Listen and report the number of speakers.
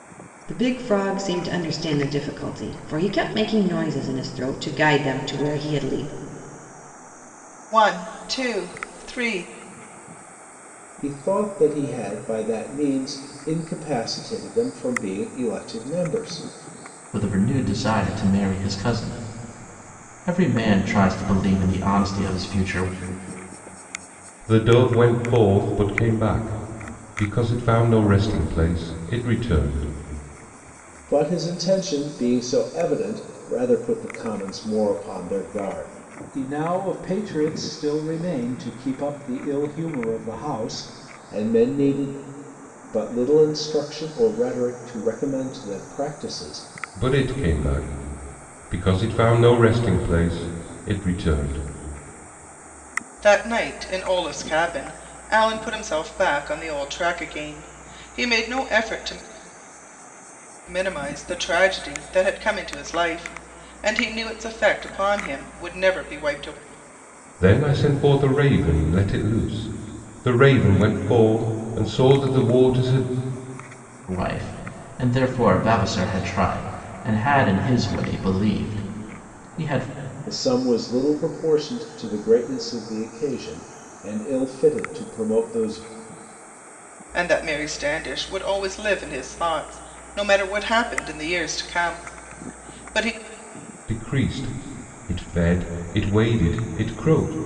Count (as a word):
five